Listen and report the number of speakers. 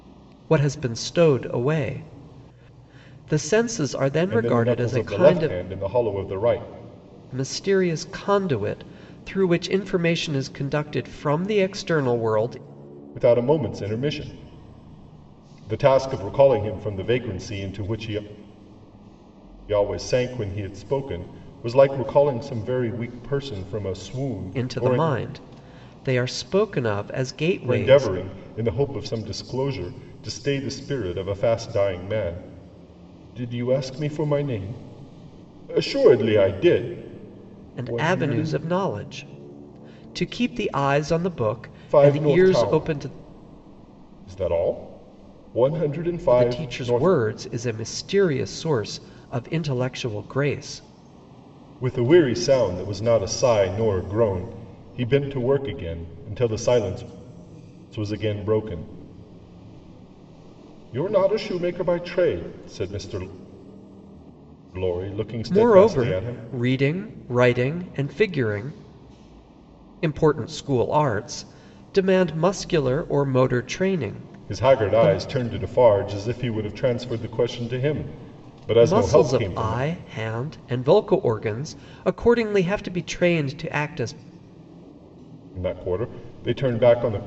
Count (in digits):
2